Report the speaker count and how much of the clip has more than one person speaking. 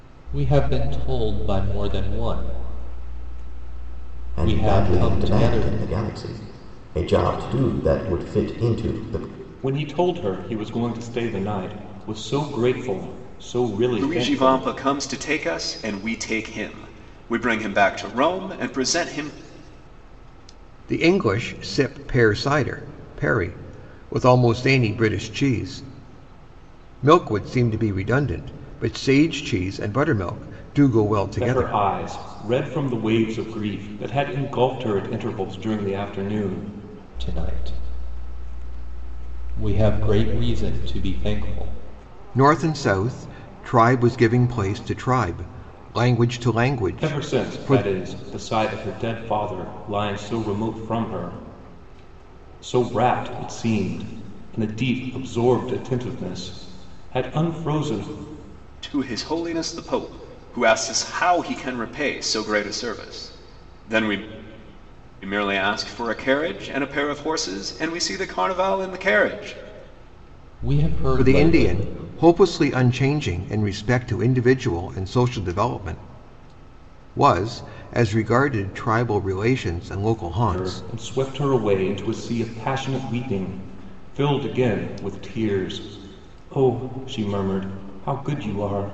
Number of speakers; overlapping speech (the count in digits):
5, about 5%